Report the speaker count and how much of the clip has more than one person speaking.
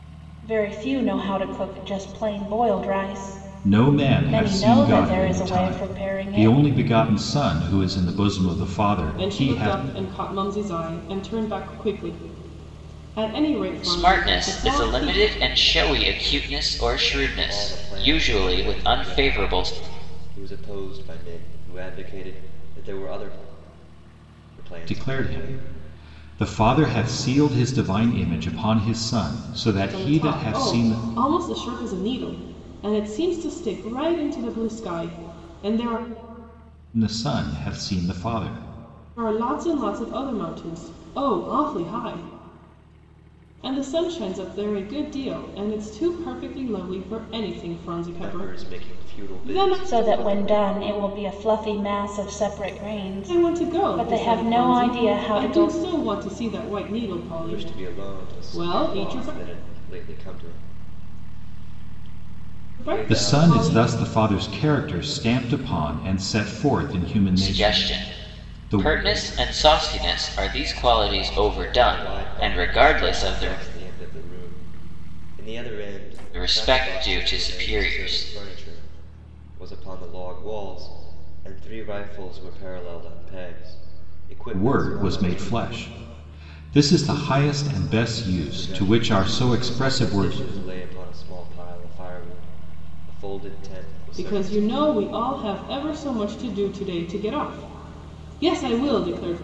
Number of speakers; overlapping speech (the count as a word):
five, about 26%